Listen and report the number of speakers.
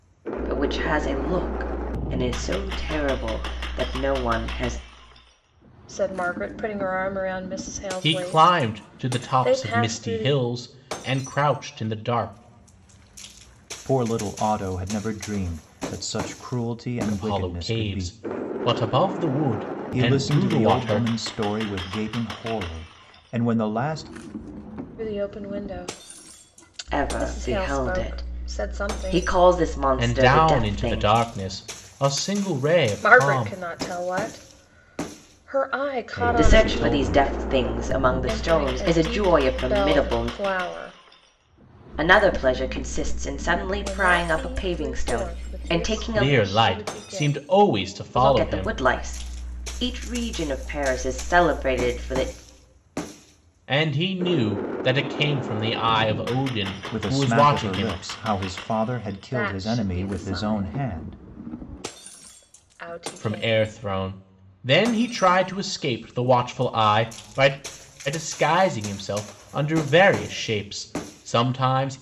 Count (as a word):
four